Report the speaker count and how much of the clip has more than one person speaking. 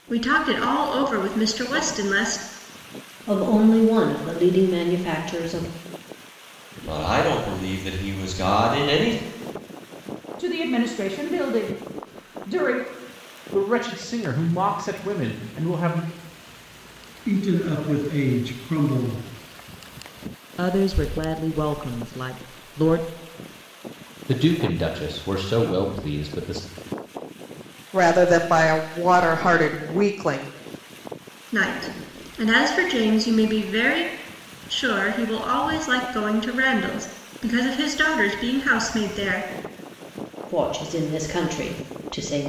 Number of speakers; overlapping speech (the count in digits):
9, no overlap